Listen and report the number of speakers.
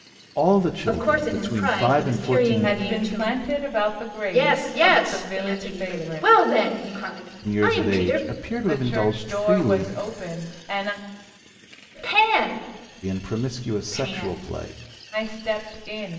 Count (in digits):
3